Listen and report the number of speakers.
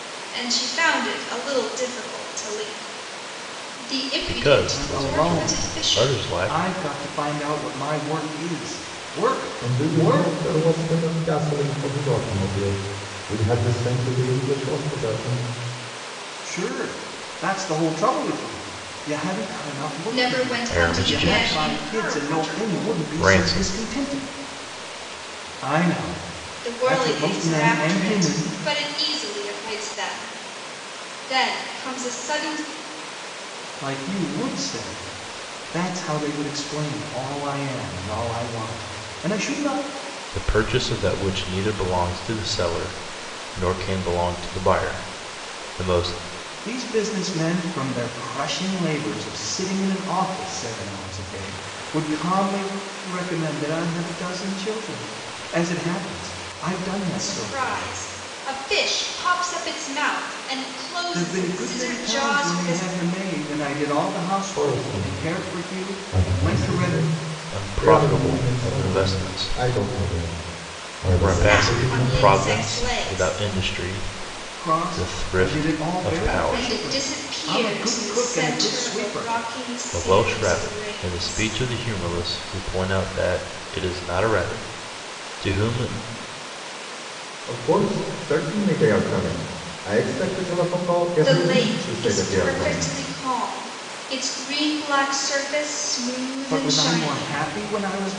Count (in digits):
4